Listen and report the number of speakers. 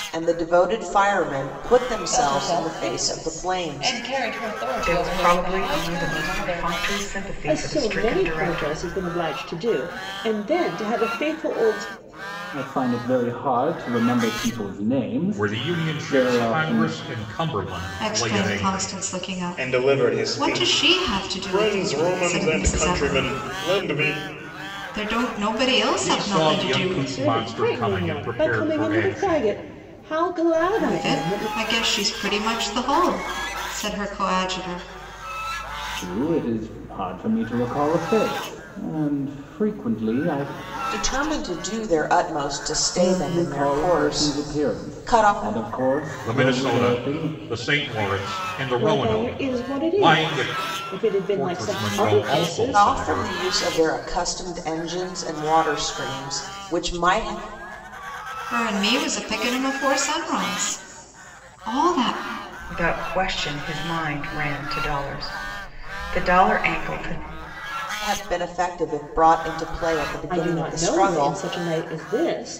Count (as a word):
eight